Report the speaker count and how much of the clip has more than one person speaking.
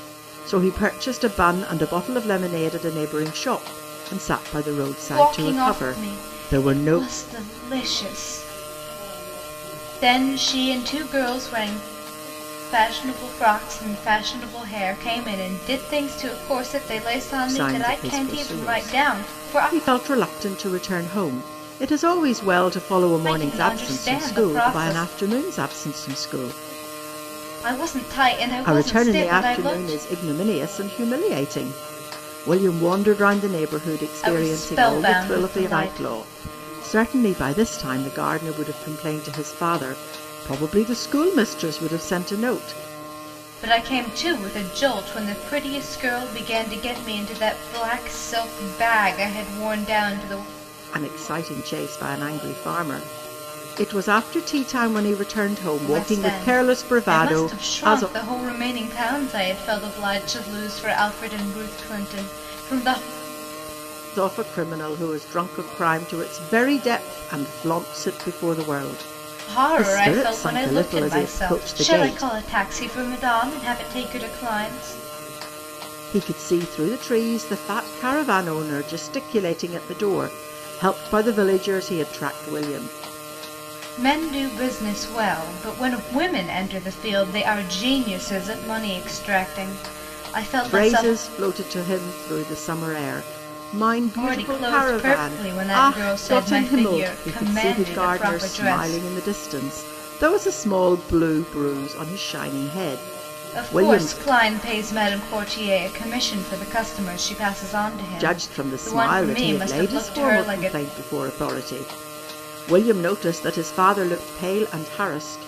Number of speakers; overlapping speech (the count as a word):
two, about 20%